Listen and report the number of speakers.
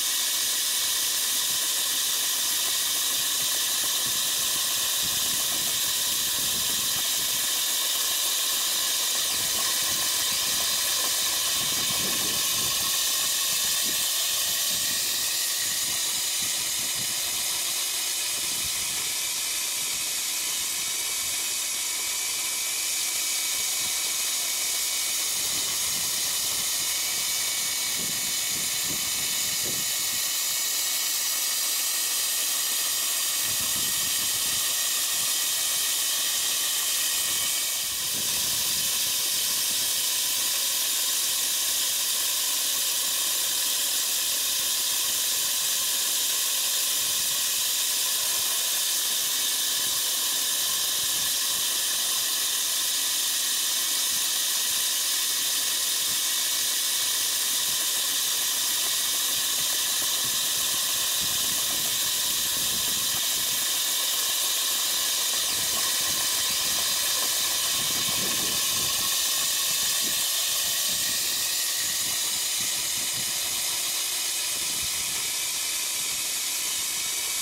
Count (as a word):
zero